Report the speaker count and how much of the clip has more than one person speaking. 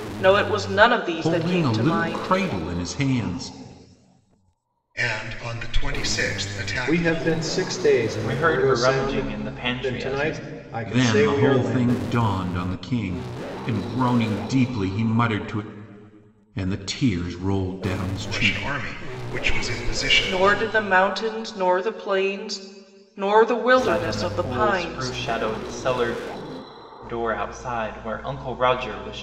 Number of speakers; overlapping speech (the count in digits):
5, about 24%